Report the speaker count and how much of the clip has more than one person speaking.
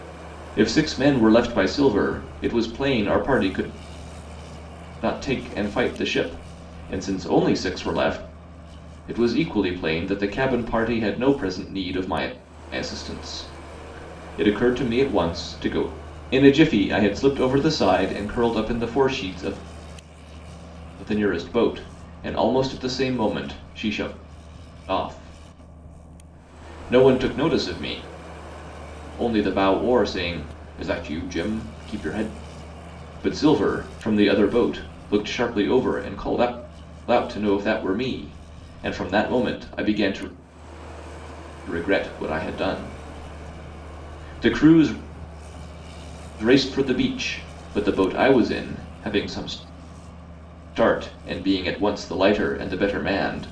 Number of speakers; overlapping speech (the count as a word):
one, no overlap